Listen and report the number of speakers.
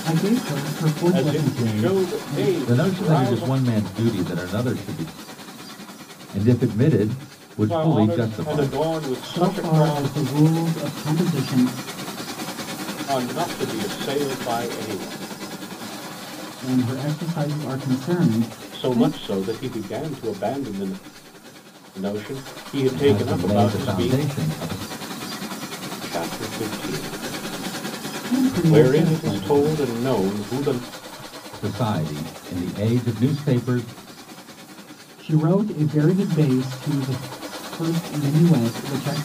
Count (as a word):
three